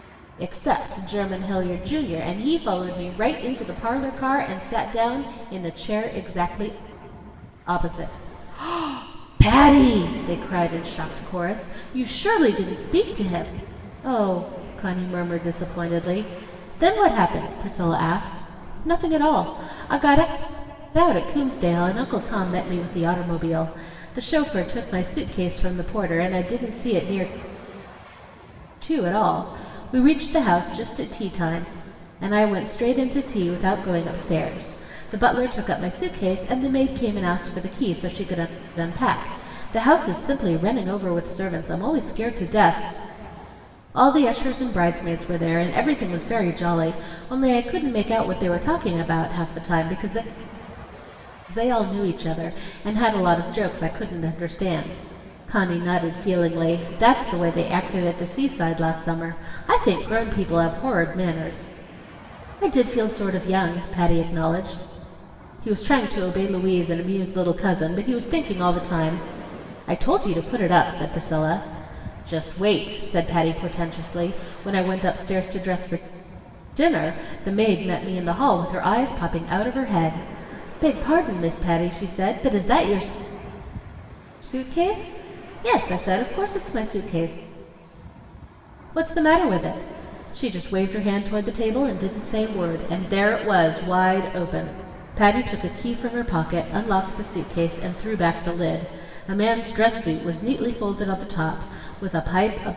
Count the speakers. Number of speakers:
1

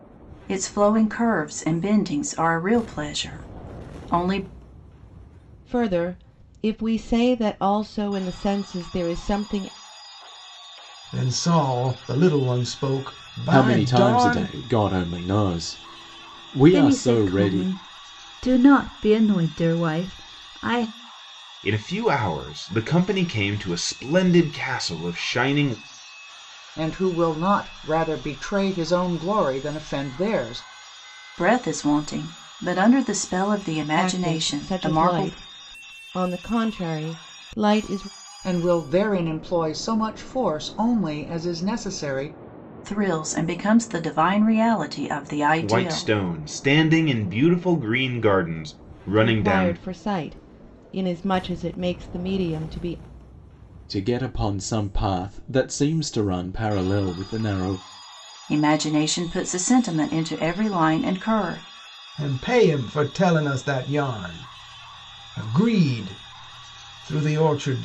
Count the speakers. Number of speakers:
7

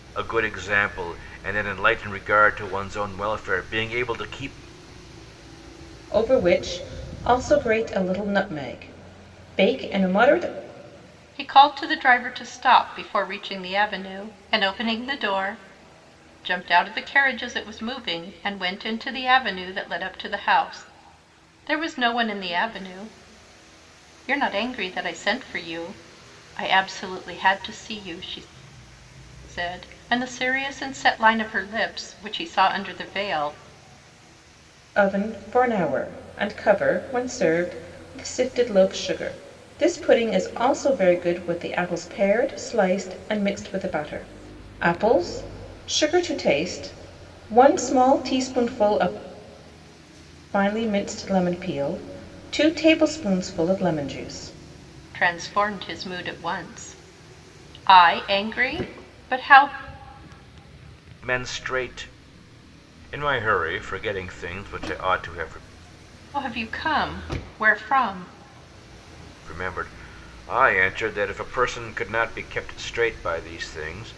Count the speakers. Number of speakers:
3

